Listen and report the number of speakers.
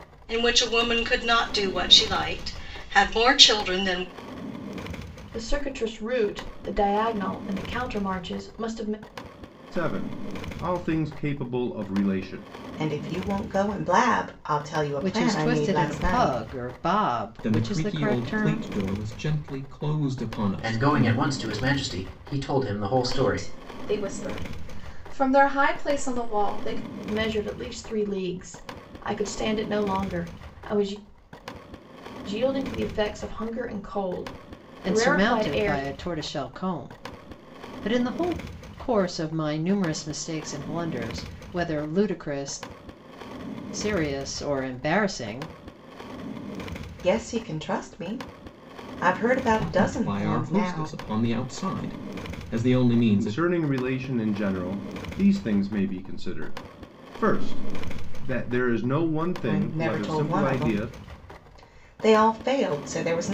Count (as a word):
eight